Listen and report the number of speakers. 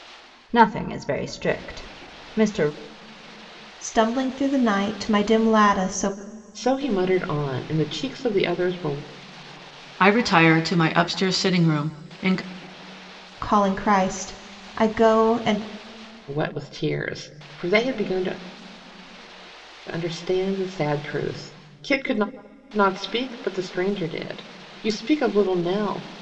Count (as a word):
four